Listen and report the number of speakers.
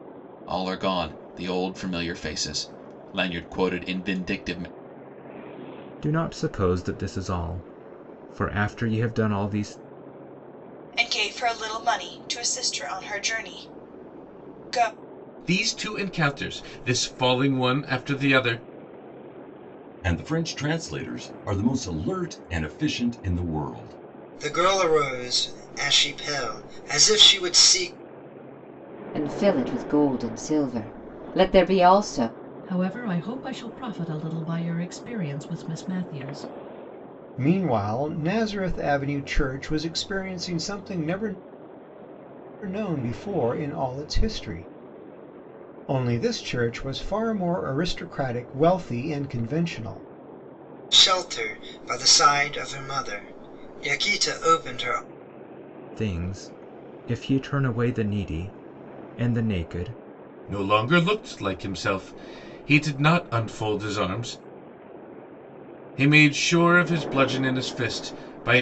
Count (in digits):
9